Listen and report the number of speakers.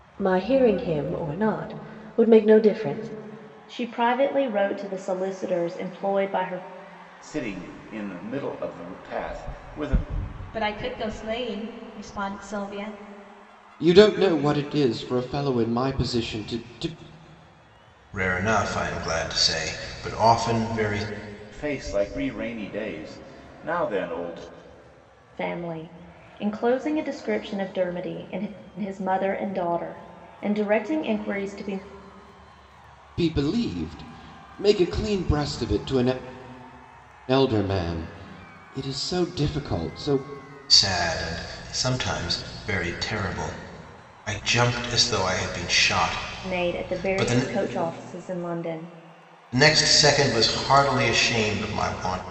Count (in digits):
6